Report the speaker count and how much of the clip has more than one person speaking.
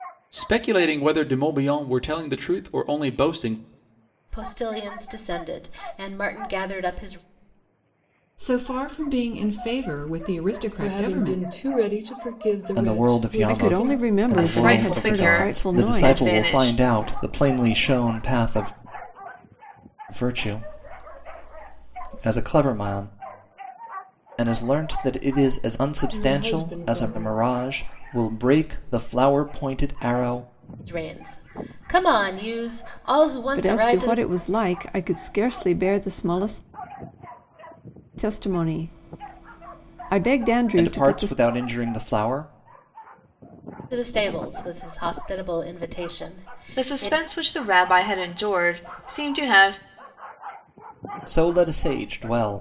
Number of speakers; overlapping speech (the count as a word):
seven, about 16%